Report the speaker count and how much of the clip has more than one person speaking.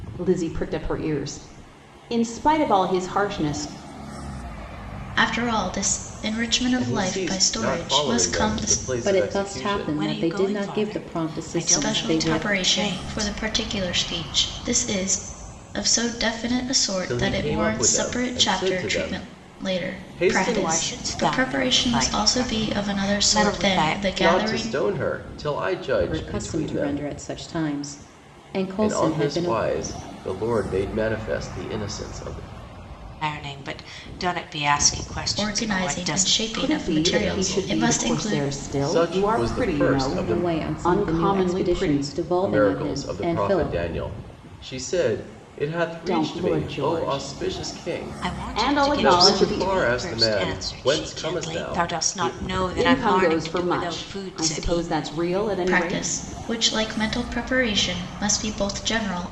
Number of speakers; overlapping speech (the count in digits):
5, about 55%